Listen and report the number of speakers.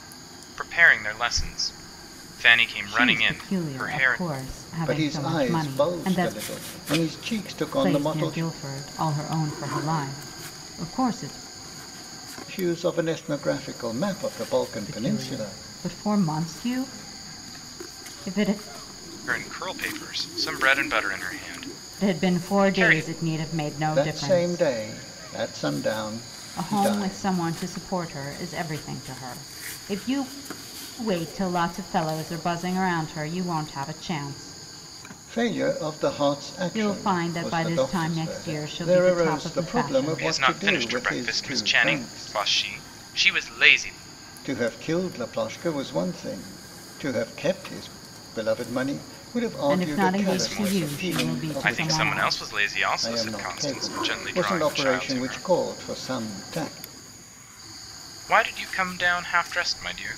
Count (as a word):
three